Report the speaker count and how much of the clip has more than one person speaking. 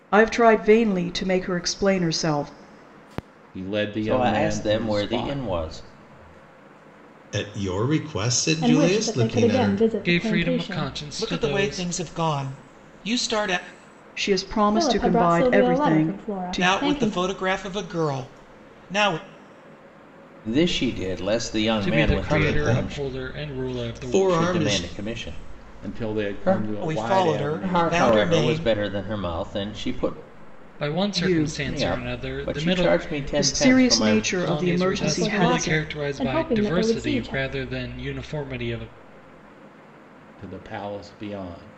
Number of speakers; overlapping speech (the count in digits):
7, about 45%